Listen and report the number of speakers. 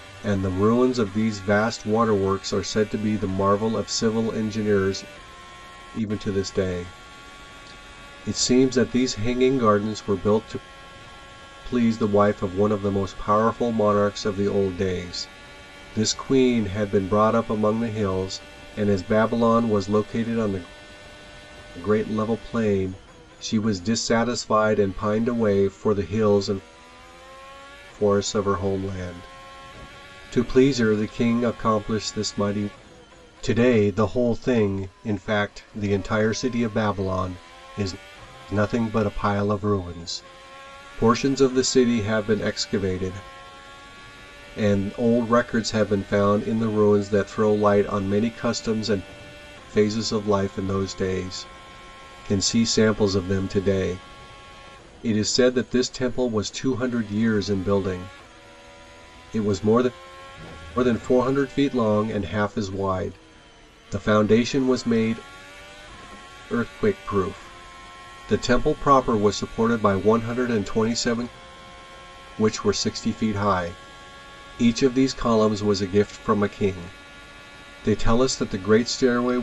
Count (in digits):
1